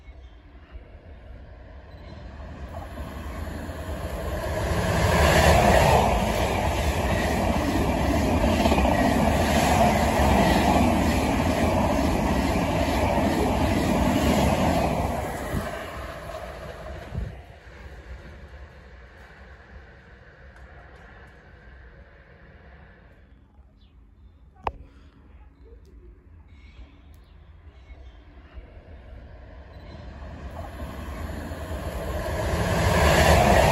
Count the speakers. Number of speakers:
0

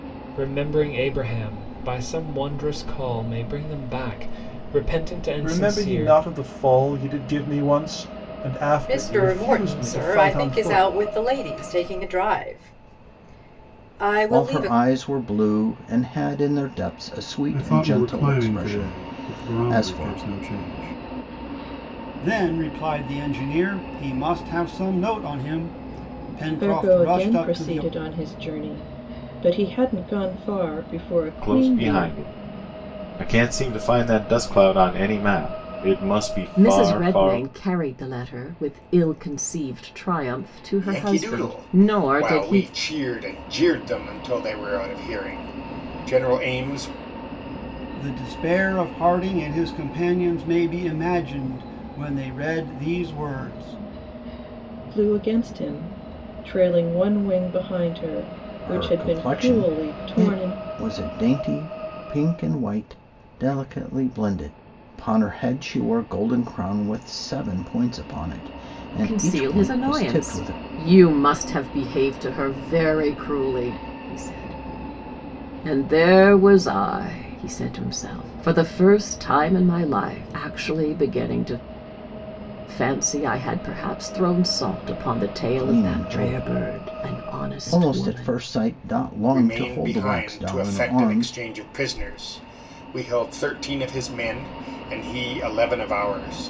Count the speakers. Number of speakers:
10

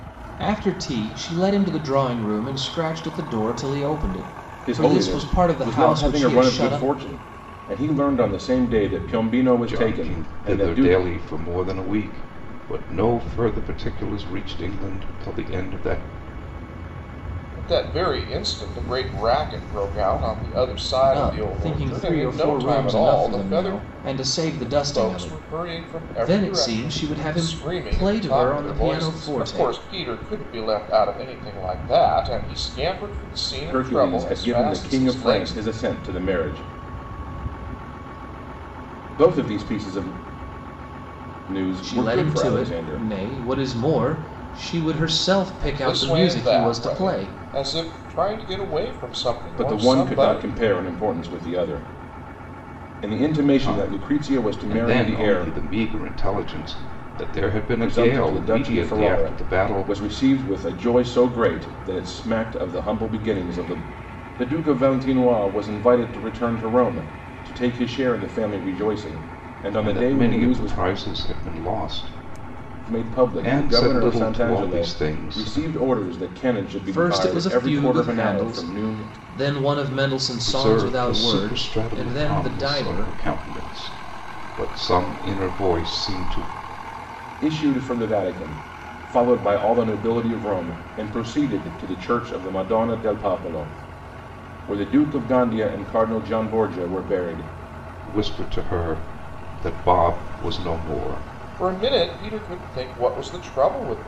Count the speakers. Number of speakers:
4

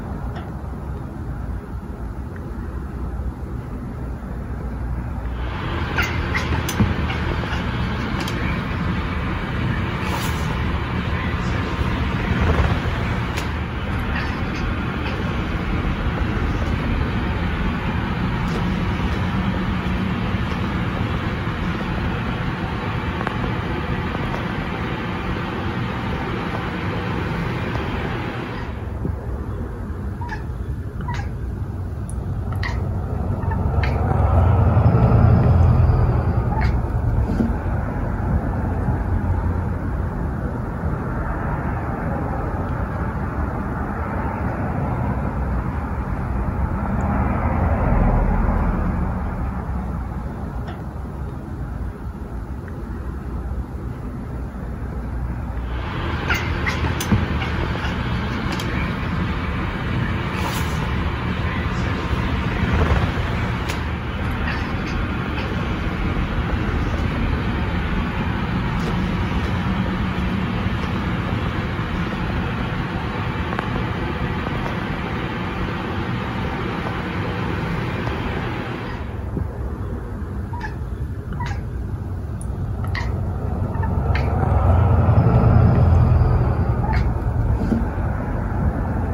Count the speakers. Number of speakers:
0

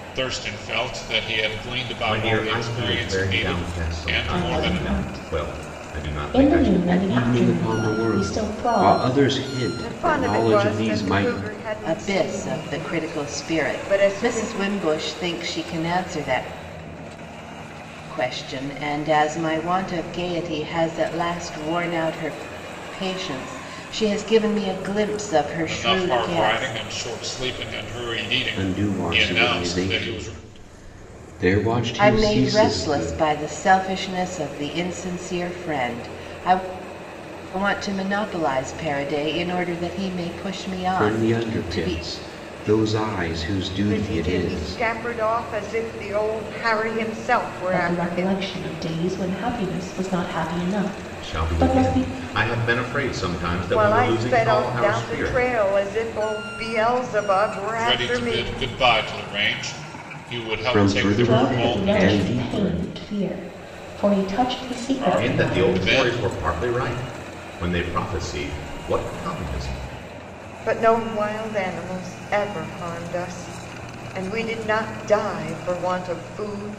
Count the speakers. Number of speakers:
6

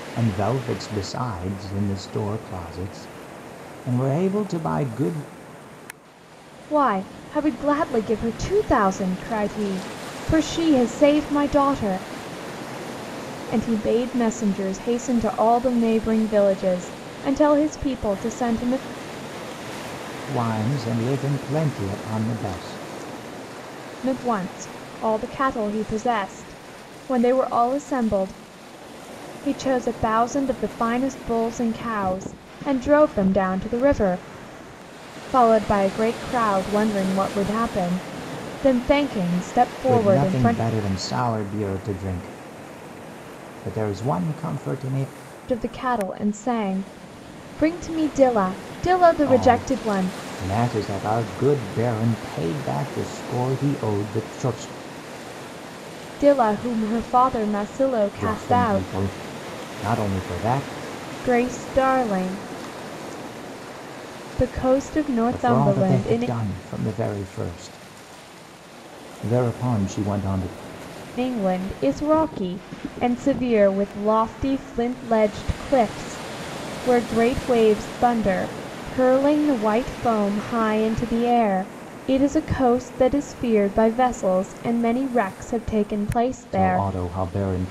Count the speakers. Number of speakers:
2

